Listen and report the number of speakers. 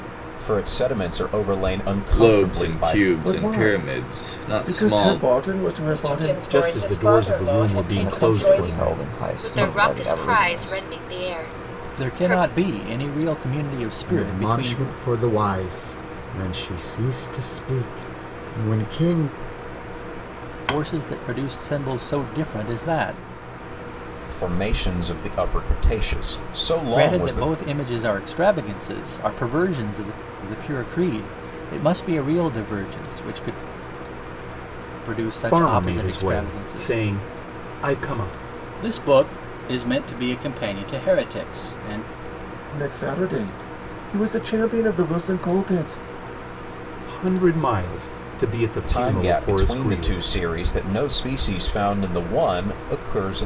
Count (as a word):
nine